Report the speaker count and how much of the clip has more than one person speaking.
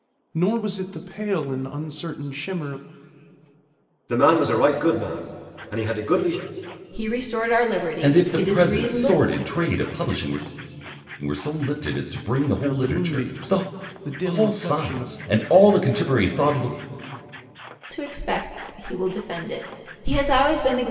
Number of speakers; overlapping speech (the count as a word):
four, about 15%